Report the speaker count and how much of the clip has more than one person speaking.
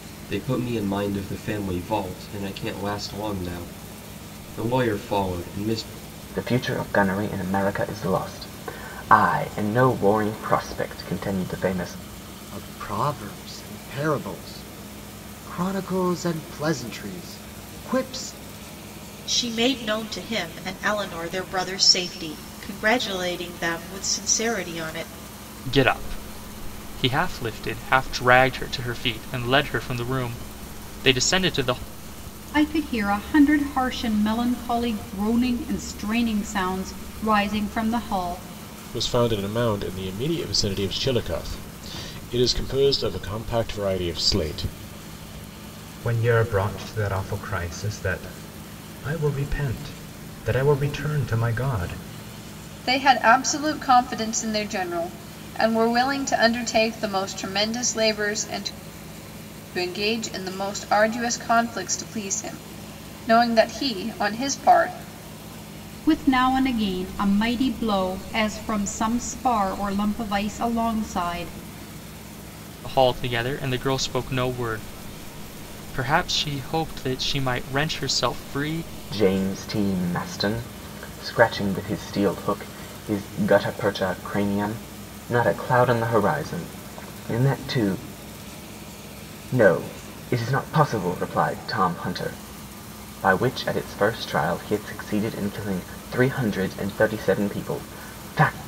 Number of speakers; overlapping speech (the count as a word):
nine, no overlap